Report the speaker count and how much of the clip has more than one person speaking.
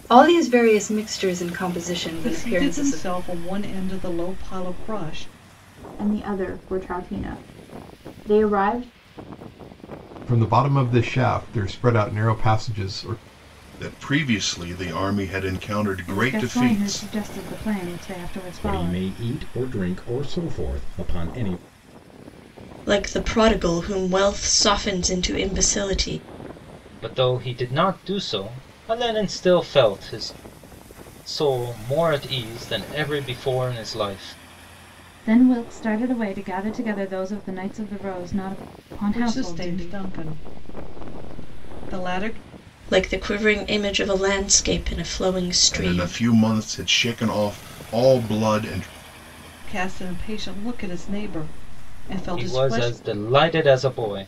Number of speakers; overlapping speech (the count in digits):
9, about 8%